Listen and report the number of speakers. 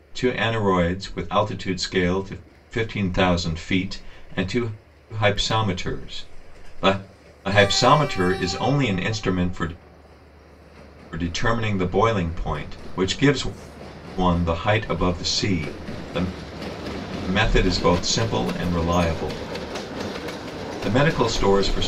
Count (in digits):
1